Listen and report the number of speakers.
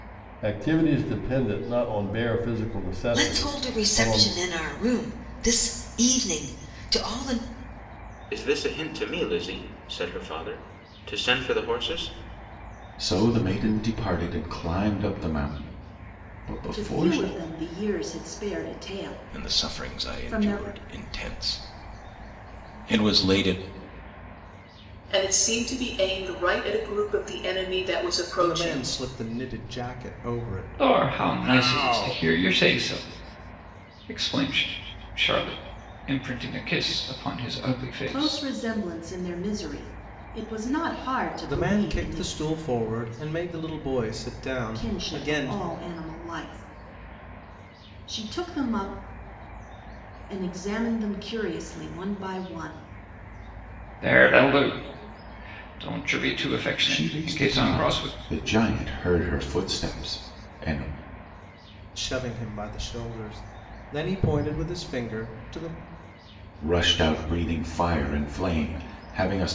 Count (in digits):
9